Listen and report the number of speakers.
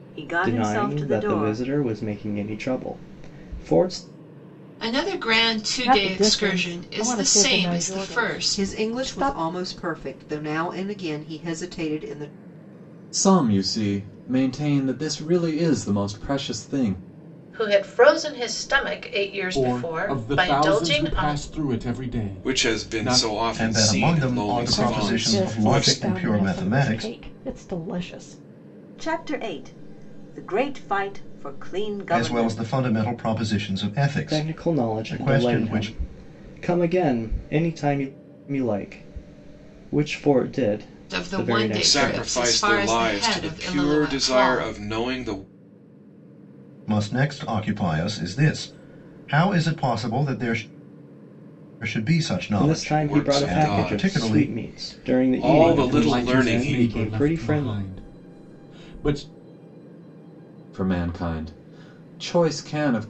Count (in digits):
10